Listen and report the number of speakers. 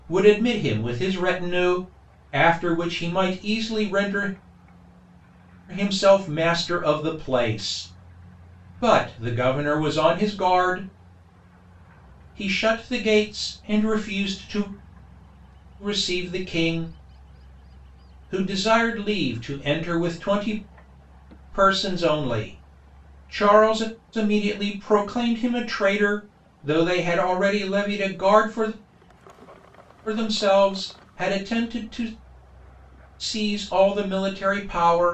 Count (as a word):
one